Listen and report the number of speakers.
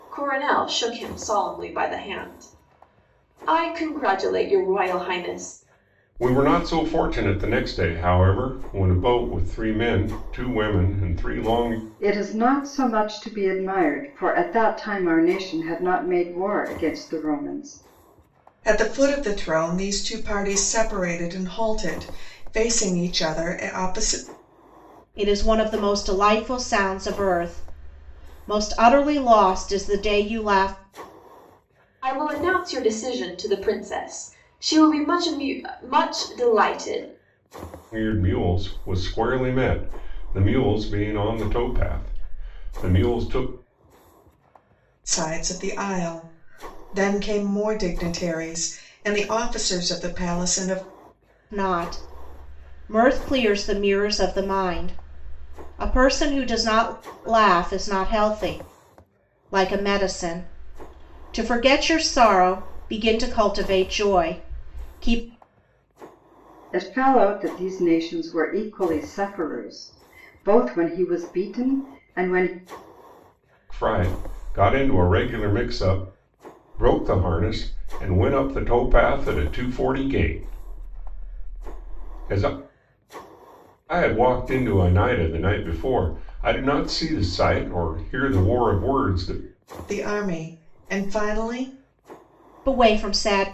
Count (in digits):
5